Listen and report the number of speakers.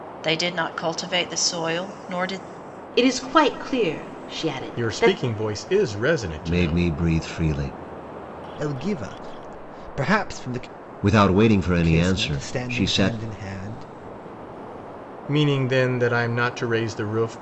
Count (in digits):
5